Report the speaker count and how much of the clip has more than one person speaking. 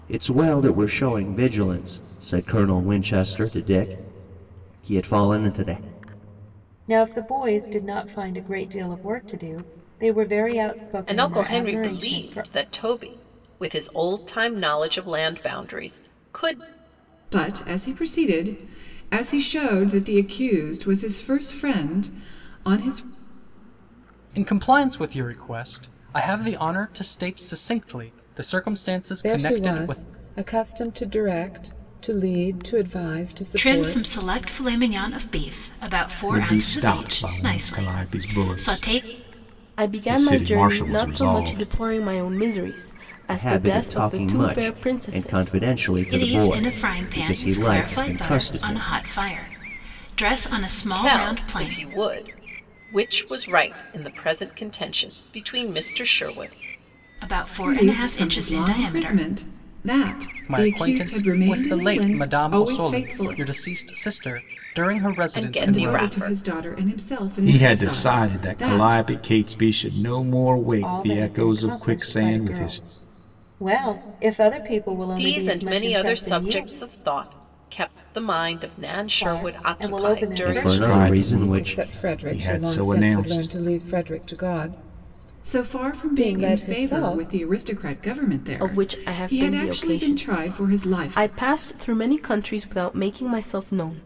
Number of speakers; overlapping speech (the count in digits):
9, about 36%